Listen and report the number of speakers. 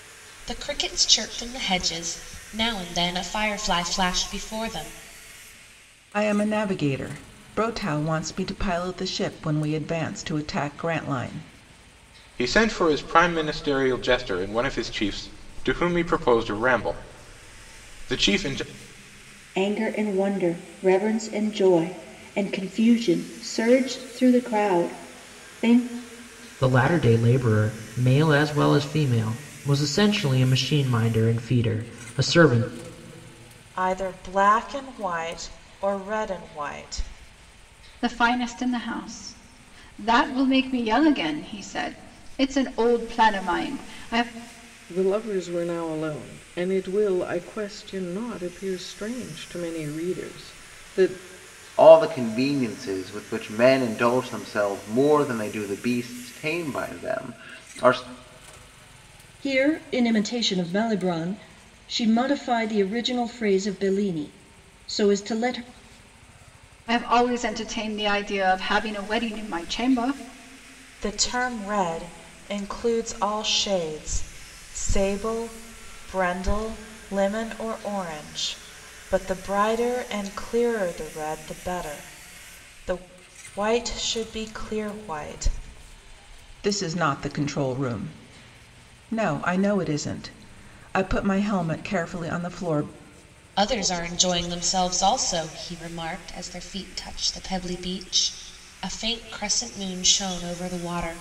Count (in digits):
10